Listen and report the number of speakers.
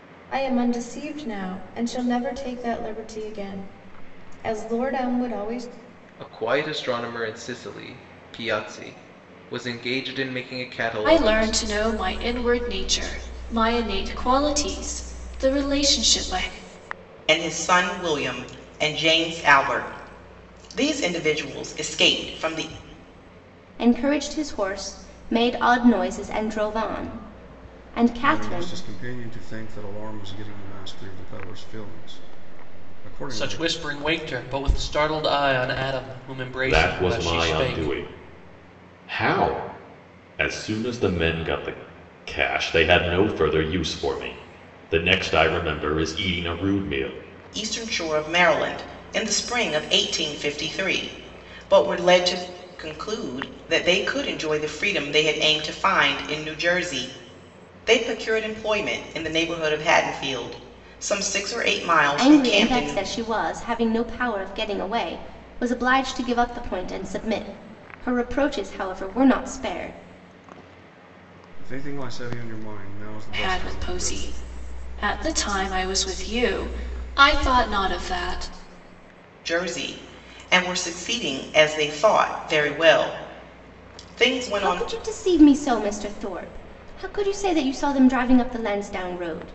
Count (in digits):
8